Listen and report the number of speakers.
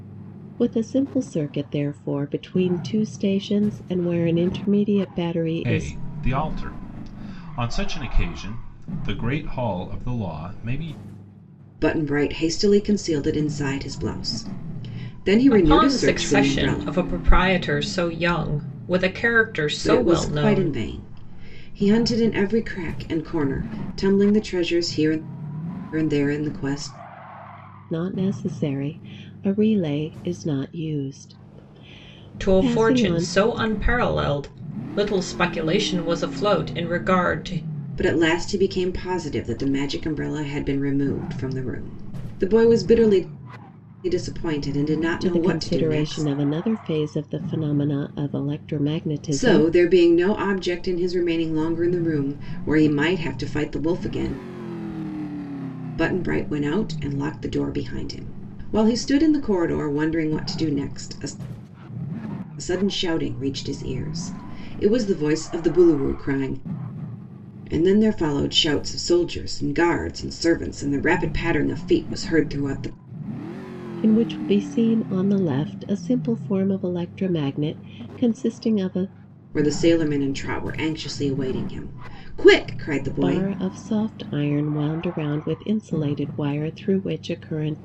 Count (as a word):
four